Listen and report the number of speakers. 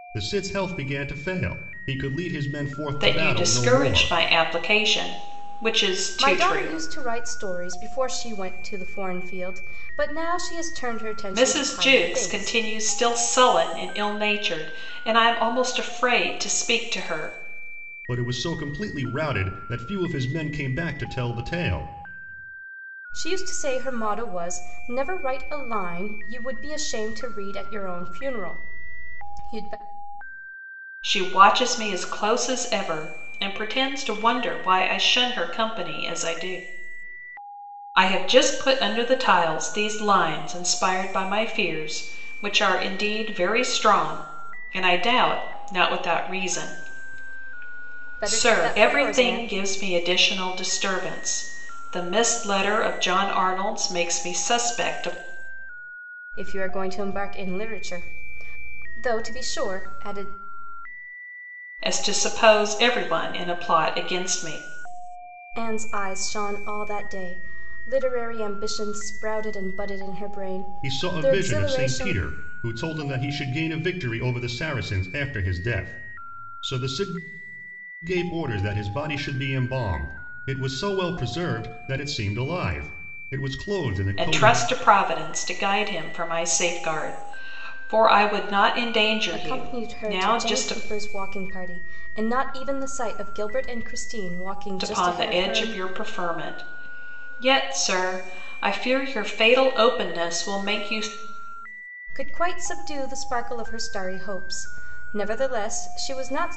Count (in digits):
3